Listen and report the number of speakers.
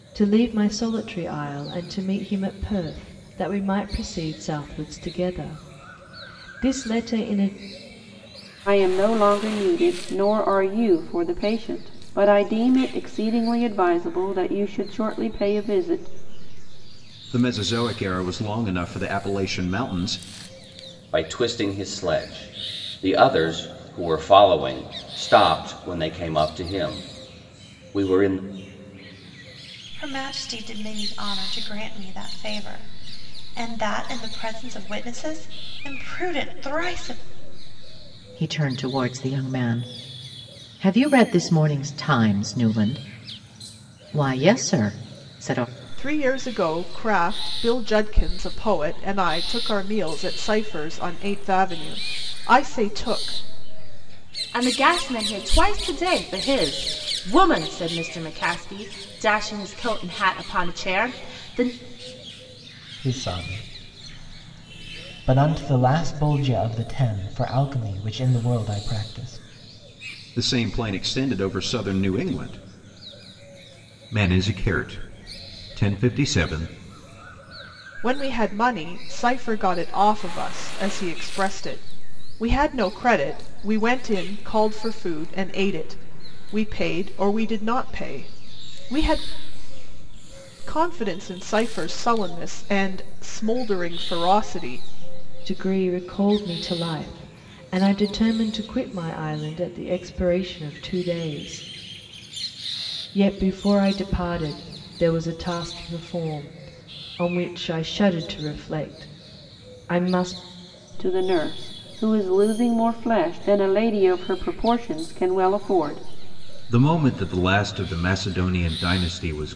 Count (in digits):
9